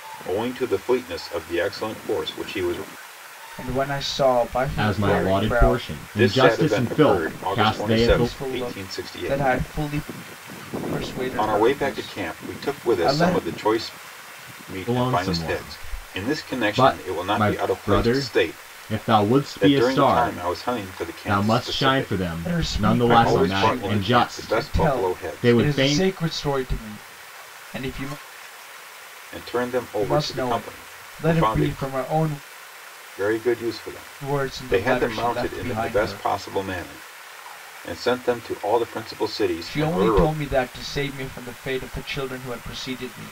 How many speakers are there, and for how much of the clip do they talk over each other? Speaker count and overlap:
3, about 46%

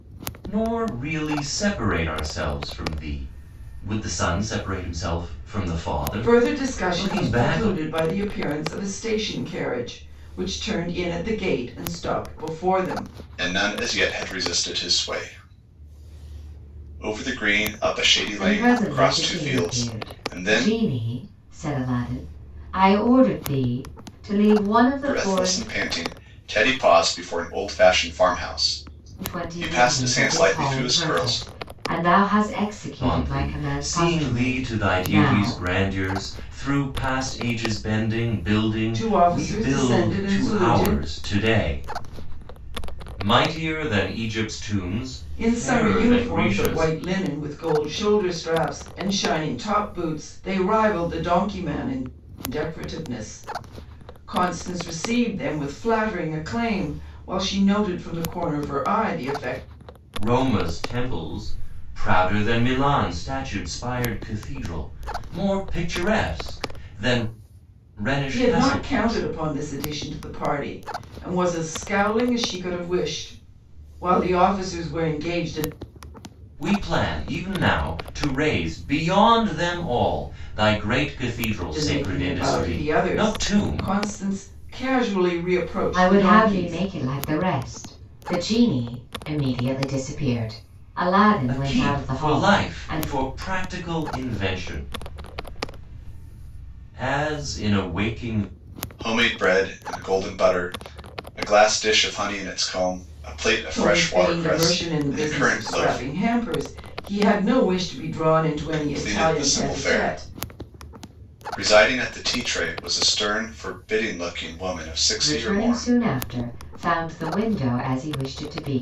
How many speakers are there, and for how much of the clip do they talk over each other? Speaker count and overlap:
4, about 20%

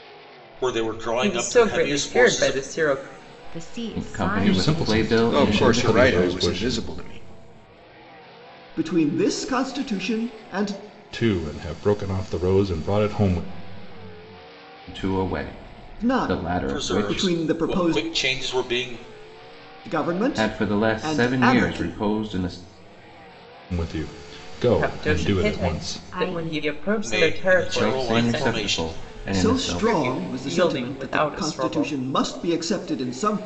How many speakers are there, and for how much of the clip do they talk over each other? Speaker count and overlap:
7, about 46%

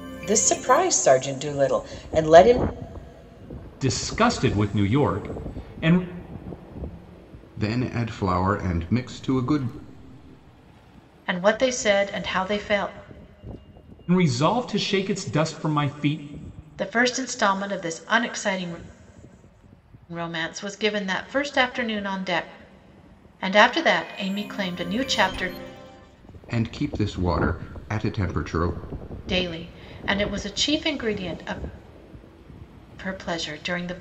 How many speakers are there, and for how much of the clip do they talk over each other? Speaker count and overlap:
4, no overlap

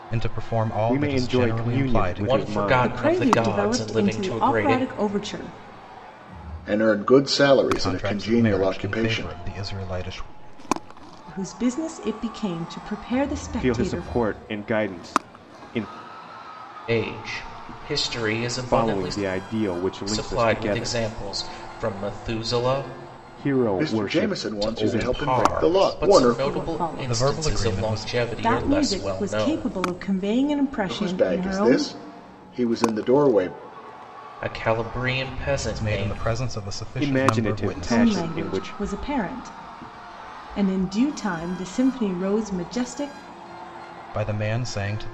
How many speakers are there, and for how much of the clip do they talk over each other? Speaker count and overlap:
5, about 38%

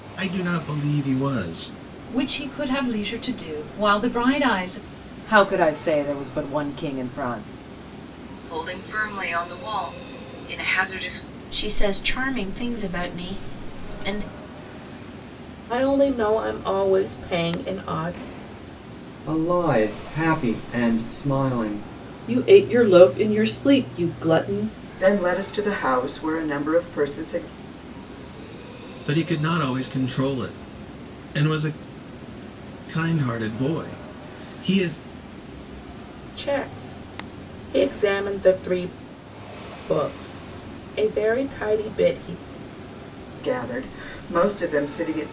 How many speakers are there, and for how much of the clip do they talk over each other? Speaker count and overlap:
9, no overlap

